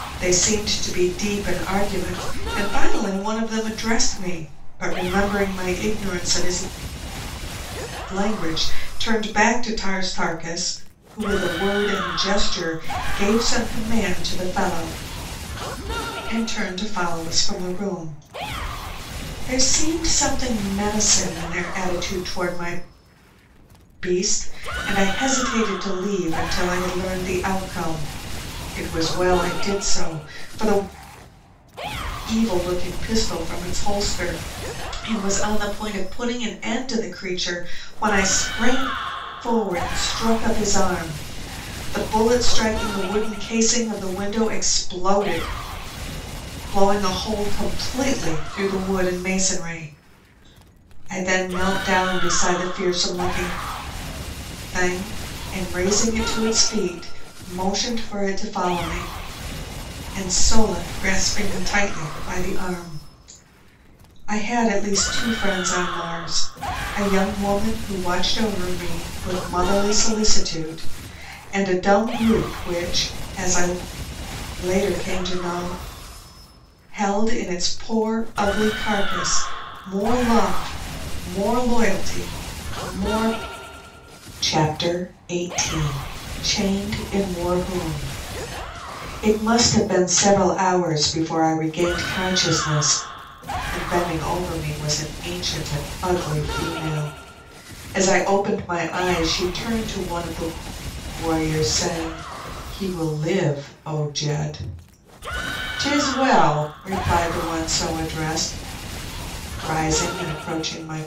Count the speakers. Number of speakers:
one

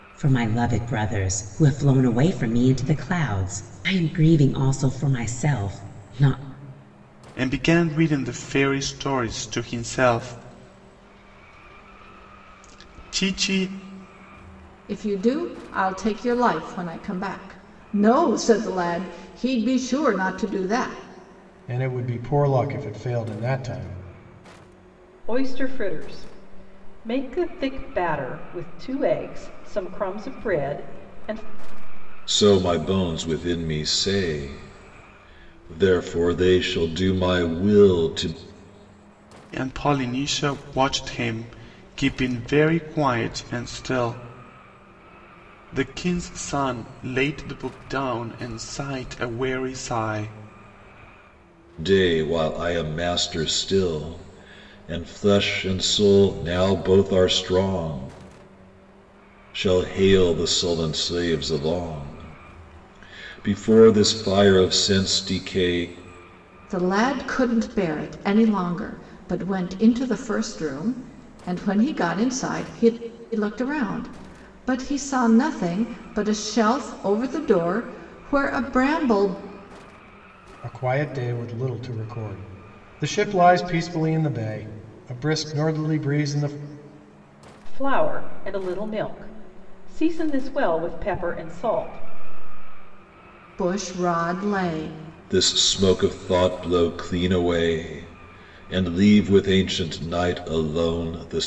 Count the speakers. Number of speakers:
six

